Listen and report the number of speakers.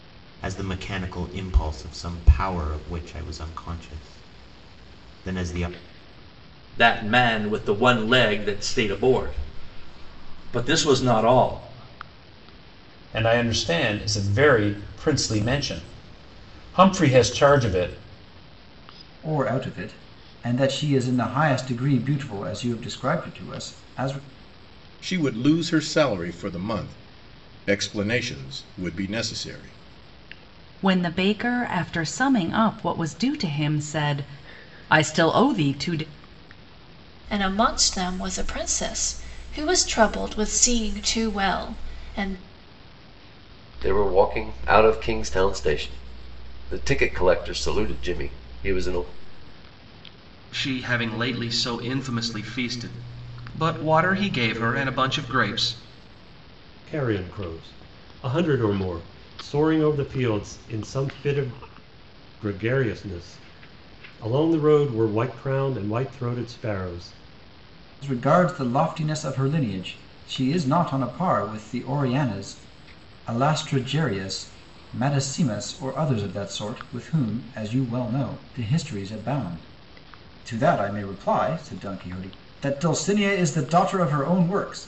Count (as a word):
ten